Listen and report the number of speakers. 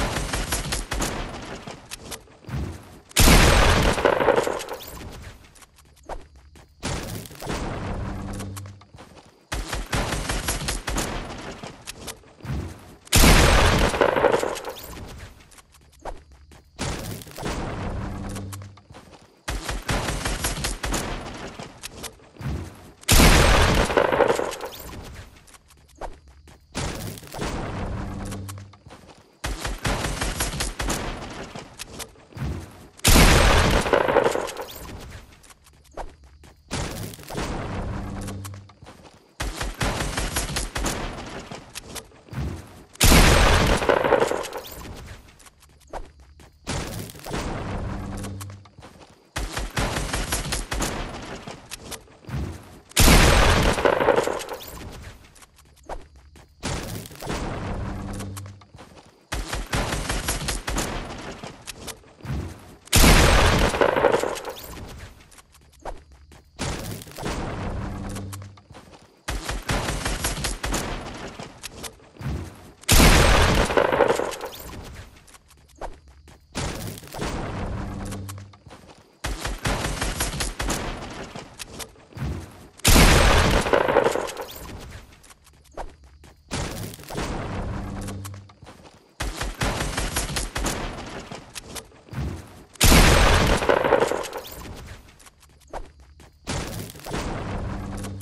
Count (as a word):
zero